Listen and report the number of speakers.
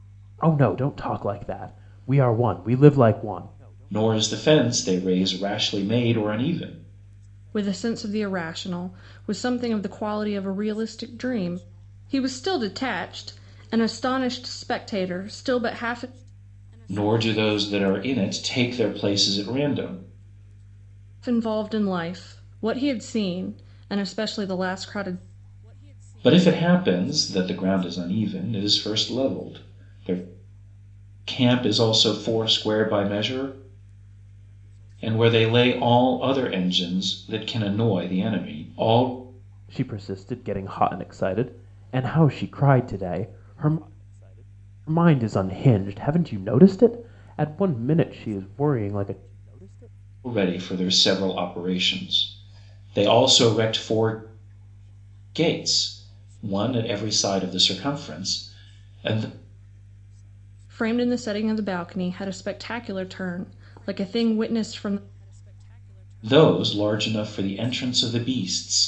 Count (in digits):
3